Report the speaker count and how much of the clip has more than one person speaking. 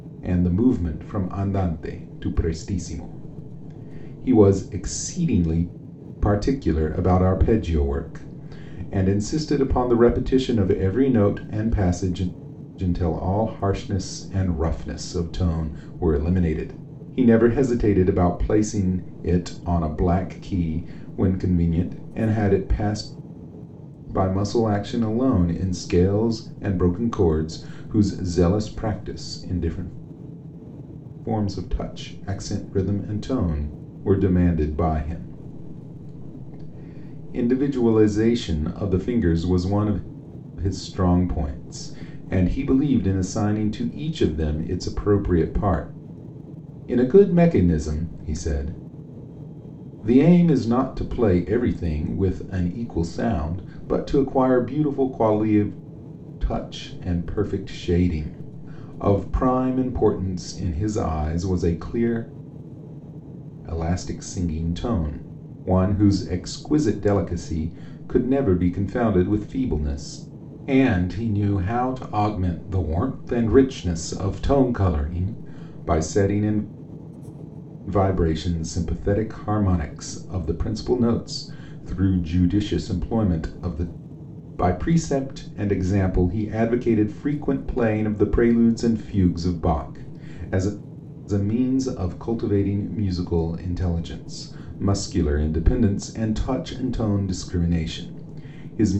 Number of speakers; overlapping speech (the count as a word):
one, no overlap